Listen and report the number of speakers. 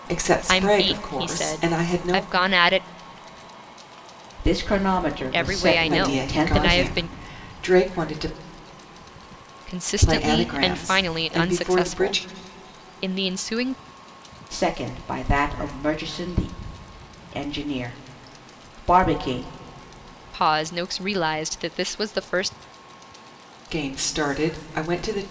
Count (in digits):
3